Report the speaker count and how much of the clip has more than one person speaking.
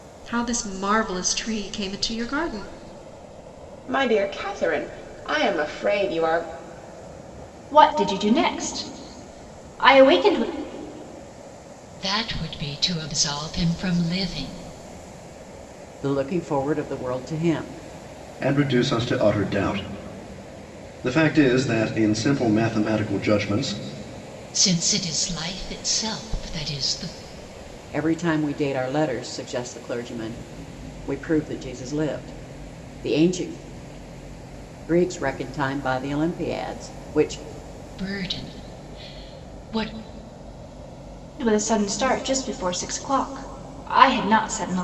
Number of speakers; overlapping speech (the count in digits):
6, no overlap